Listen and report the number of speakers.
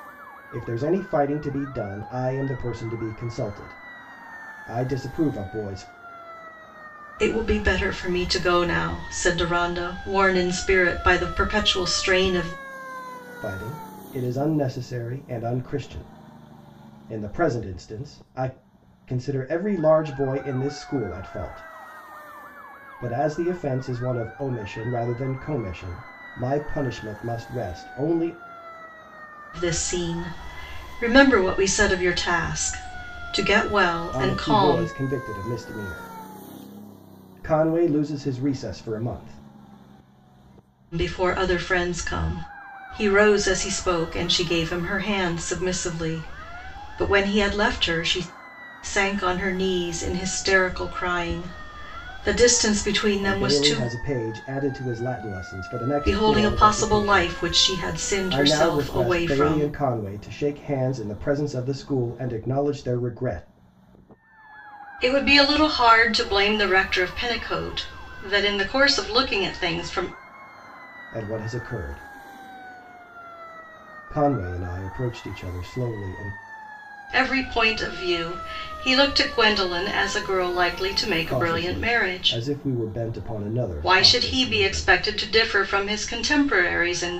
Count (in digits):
2